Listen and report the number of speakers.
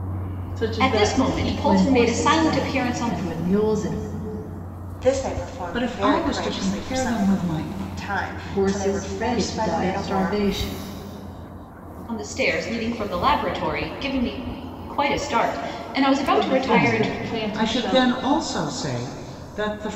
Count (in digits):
5